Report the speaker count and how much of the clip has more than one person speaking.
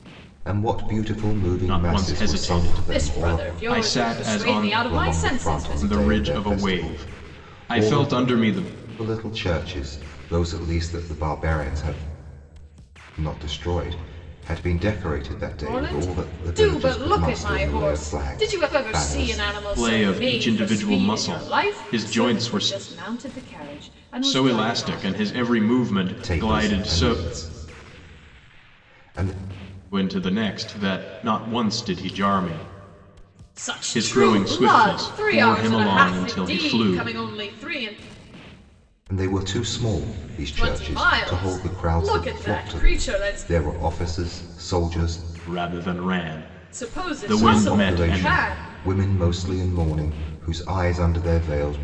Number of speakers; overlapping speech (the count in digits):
3, about 47%